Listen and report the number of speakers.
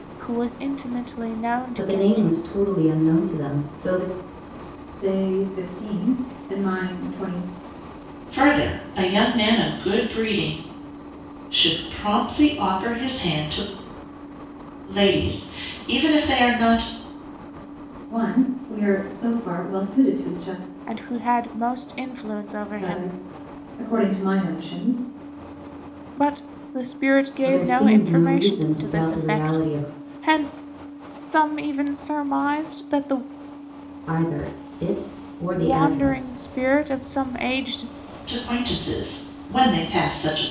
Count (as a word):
four